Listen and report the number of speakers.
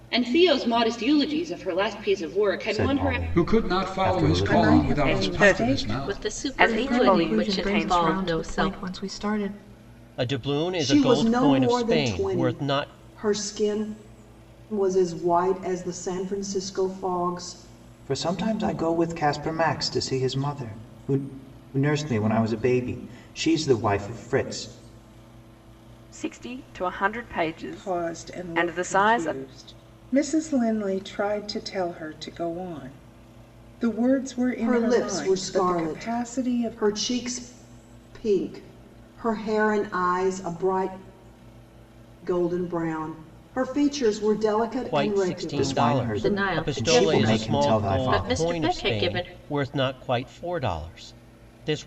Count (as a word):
nine